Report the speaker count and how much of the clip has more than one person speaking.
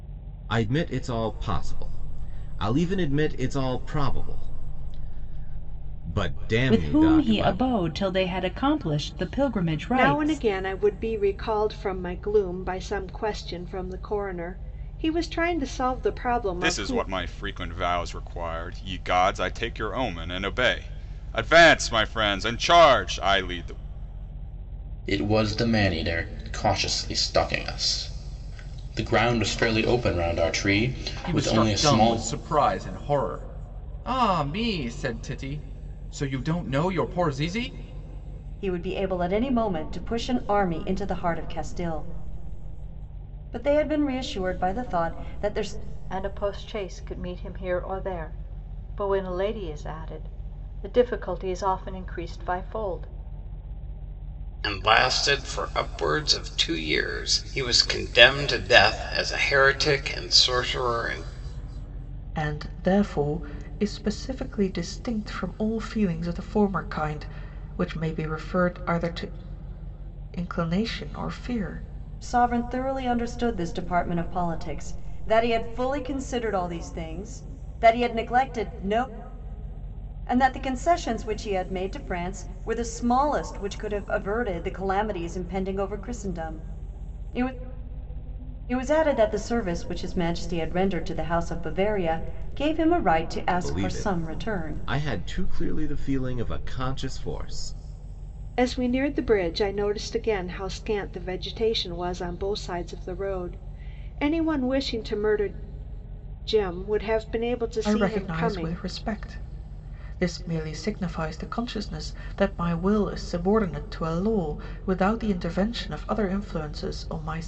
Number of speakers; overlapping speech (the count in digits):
10, about 5%